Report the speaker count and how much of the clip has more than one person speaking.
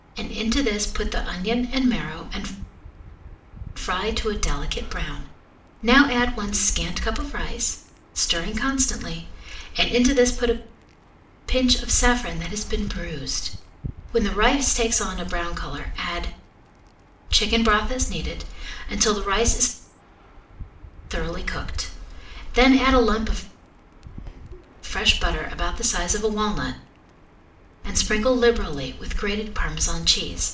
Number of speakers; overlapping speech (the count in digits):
1, no overlap